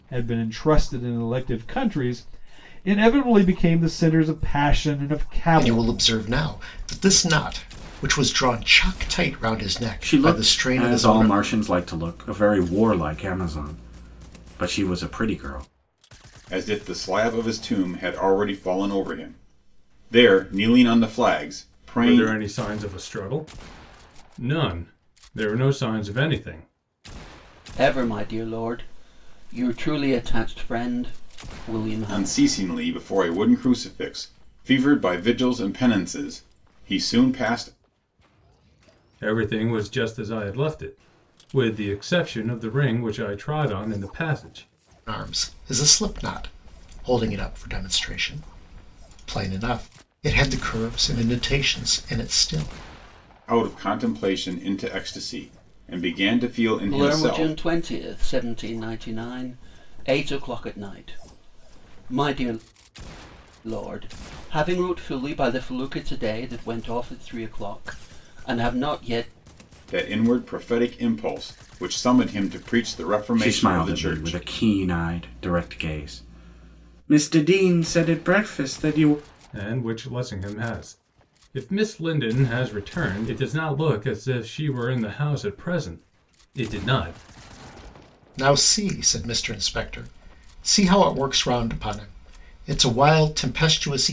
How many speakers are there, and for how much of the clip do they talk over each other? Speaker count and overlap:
6, about 5%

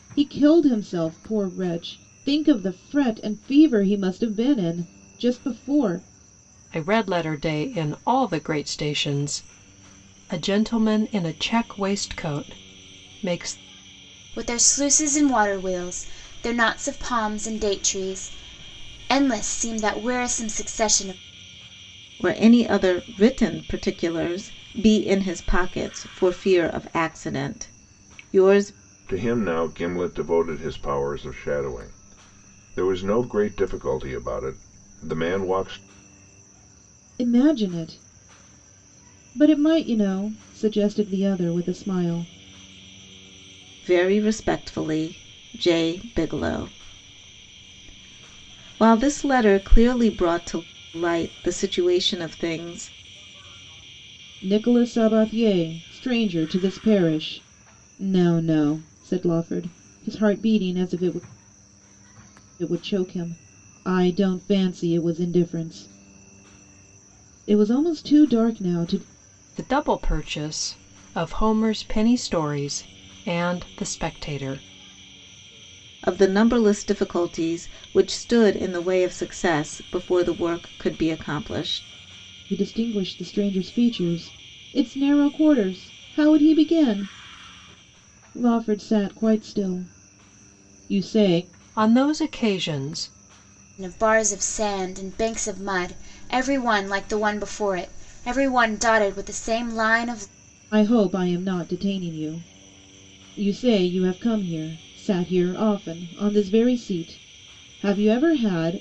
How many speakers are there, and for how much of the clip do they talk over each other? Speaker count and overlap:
5, no overlap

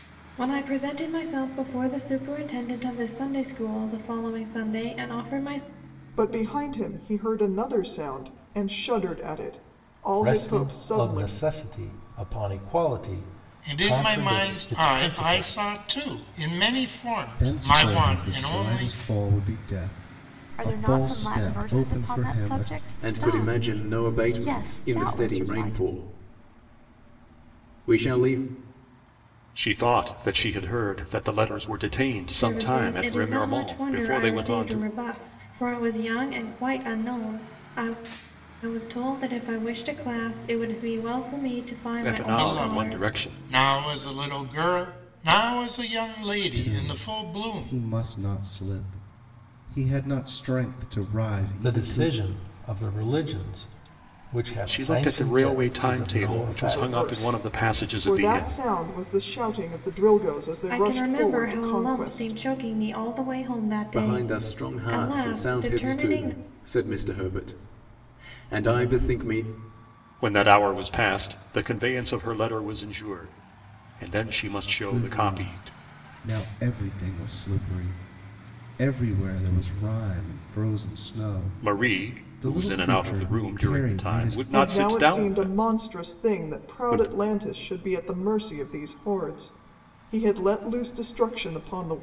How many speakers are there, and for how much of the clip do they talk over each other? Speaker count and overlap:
8, about 33%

